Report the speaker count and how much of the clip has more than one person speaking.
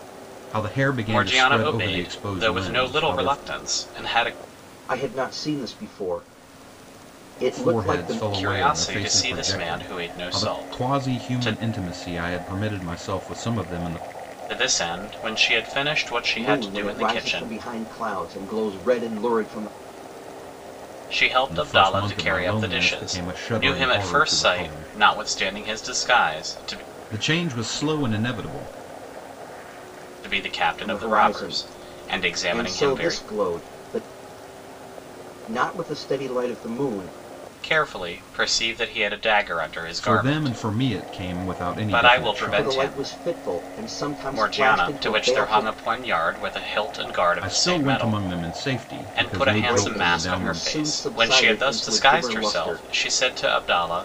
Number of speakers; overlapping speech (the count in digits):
3, about 41%